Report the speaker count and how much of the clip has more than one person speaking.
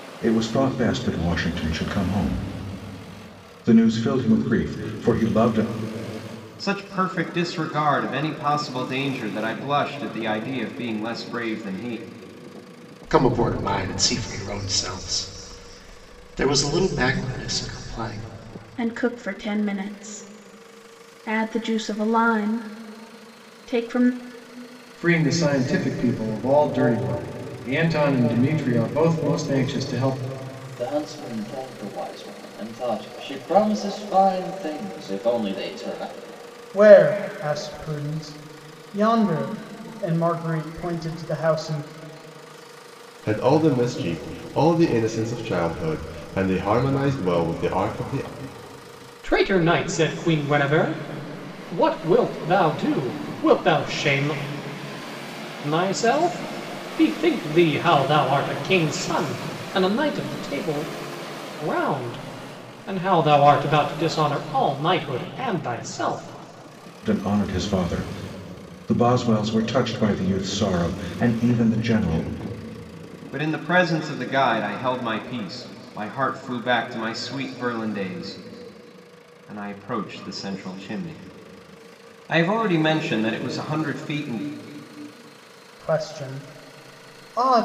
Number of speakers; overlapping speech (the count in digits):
9, no overlap